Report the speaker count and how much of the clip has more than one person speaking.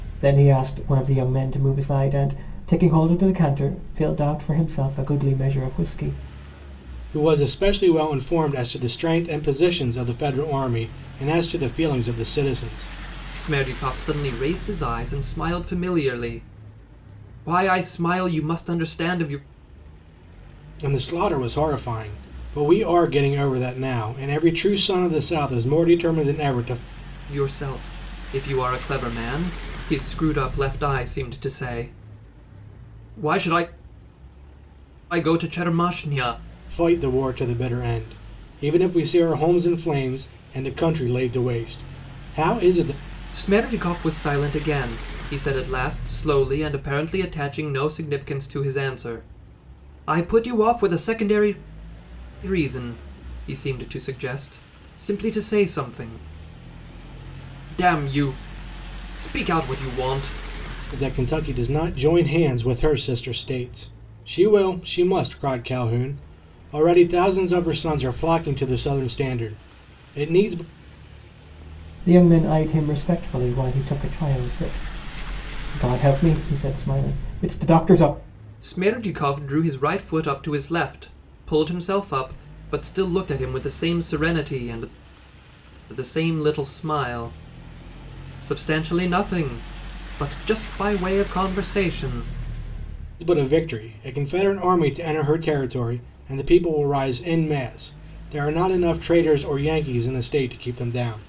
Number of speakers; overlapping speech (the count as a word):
three, no overlap